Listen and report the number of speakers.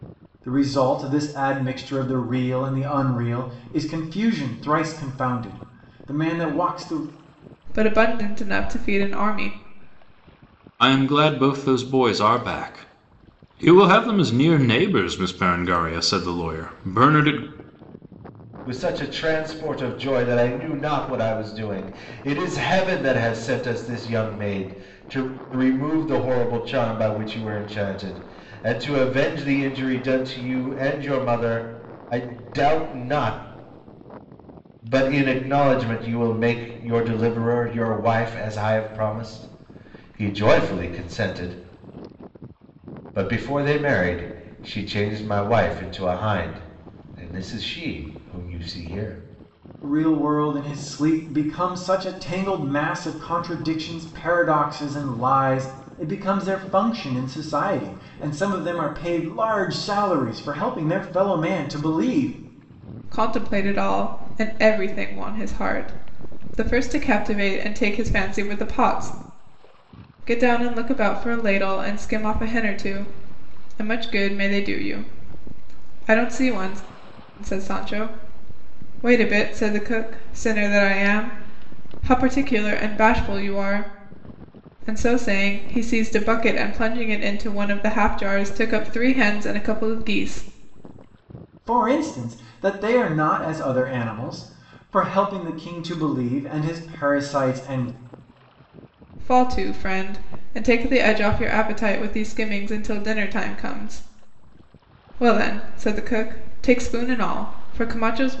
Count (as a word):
four